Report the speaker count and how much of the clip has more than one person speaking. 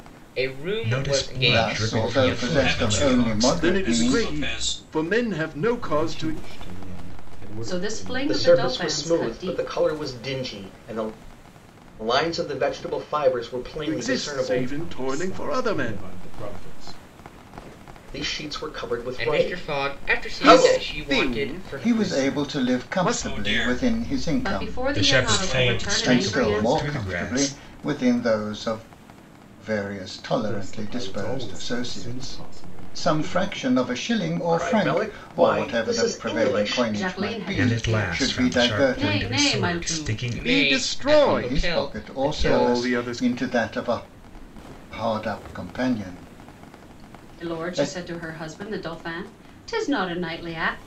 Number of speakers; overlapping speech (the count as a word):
eight, about 57%